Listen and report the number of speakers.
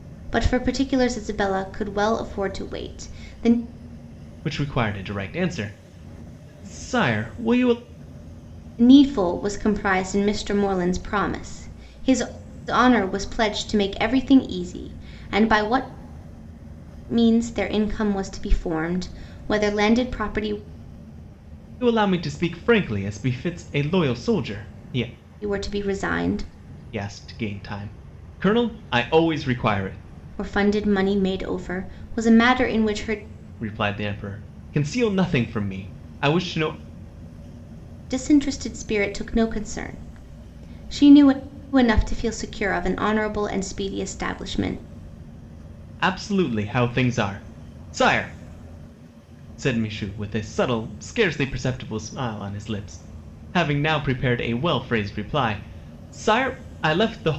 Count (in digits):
2